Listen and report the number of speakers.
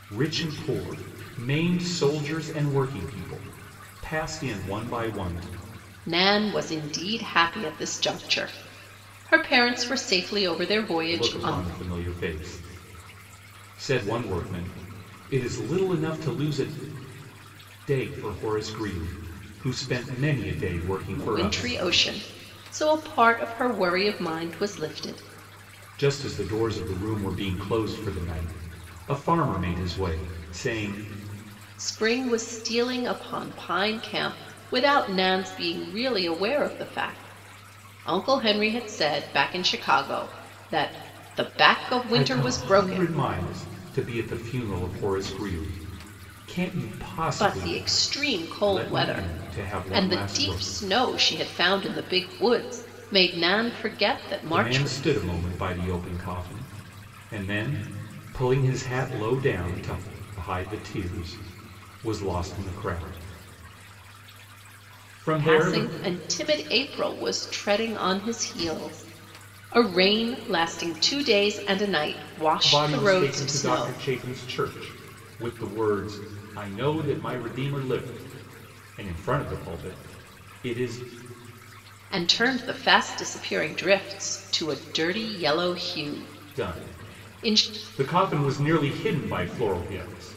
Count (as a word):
two